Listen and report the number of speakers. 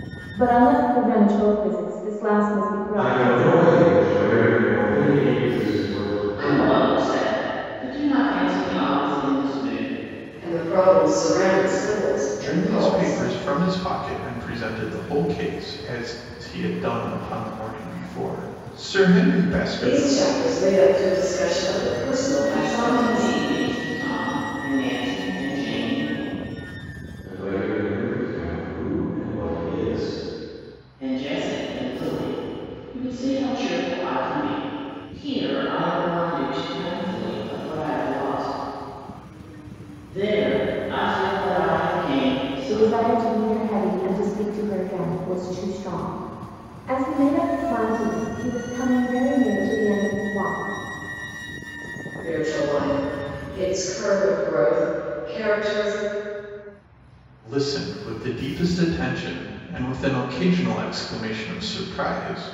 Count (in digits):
5